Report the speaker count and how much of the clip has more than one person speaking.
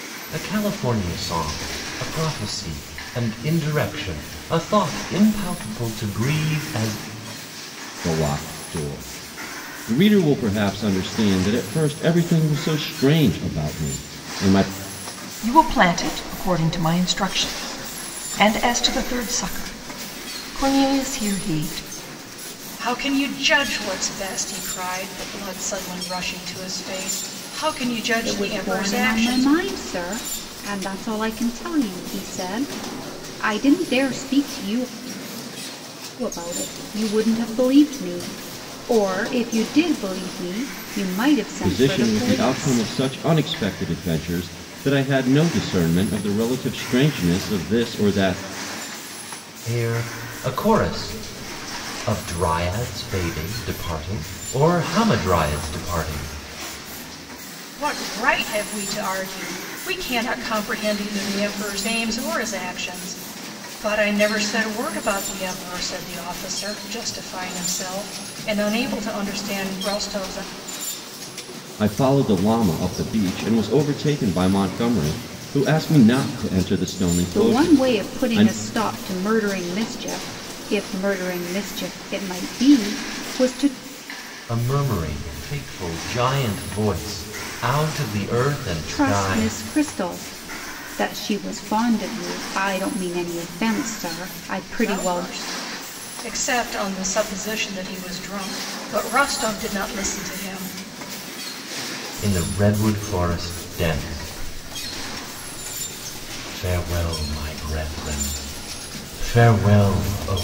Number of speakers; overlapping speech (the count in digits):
5, about 5%